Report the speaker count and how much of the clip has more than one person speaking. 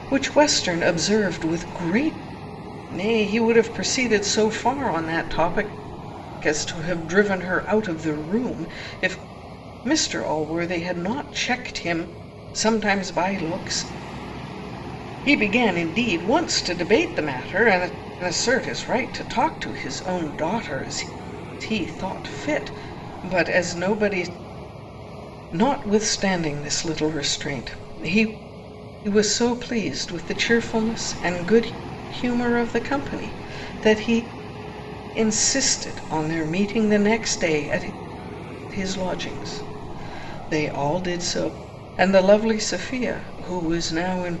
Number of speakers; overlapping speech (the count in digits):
1, no overlap